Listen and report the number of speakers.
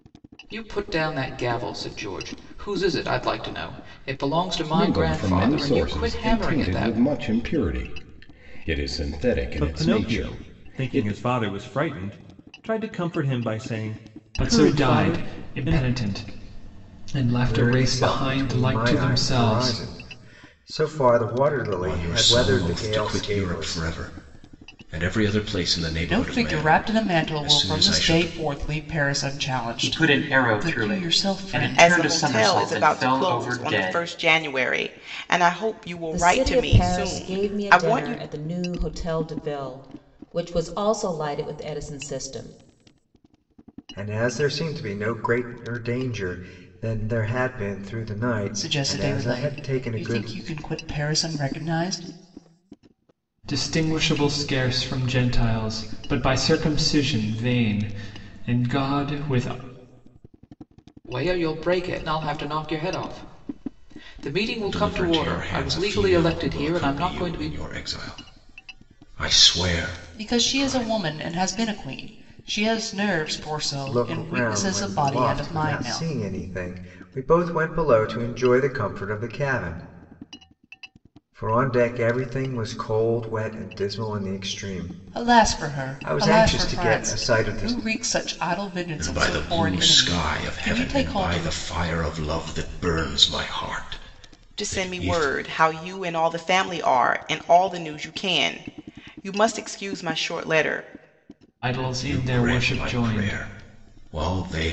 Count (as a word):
ten